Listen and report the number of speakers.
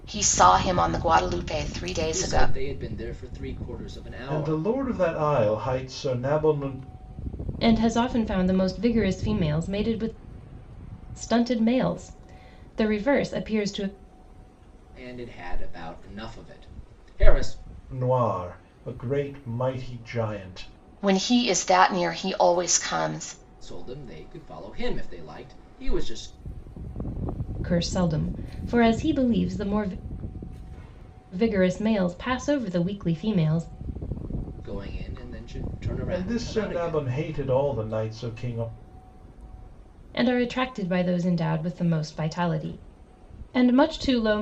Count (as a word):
four